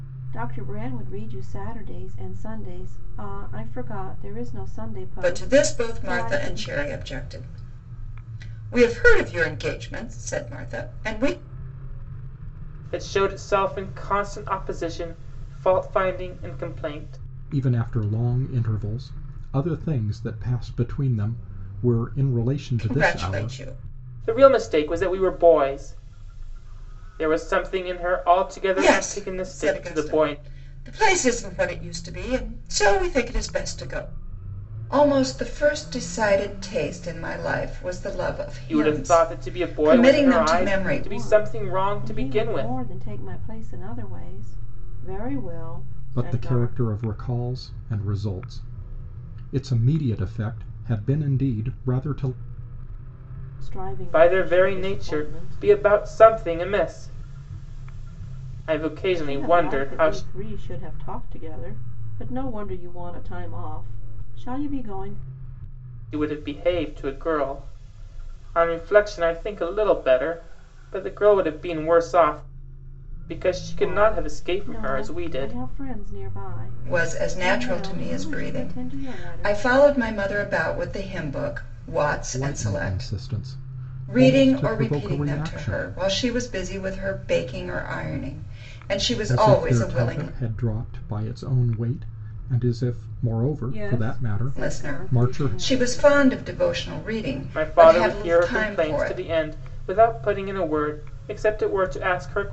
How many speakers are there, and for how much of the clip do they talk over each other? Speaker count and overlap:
4, about 24%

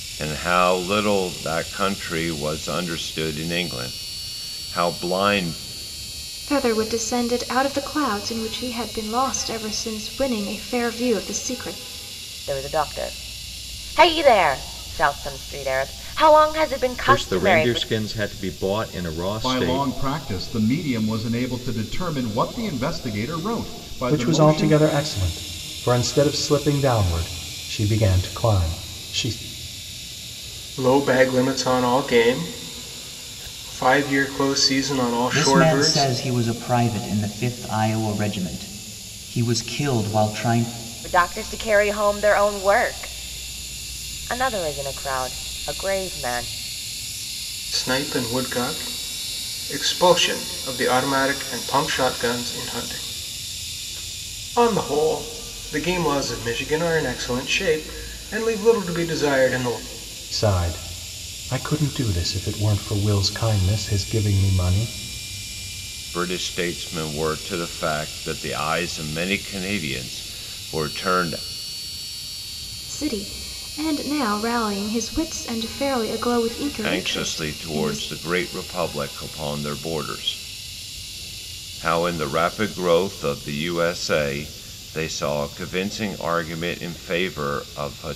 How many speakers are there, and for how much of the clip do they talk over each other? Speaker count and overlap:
8, about 5%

